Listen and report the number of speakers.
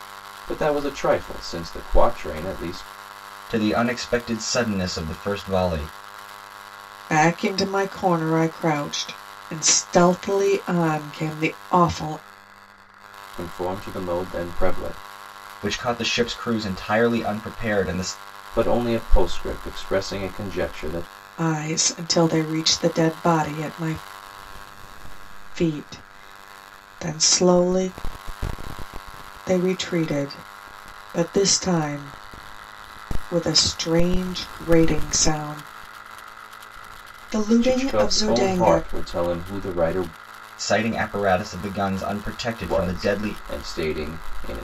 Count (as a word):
three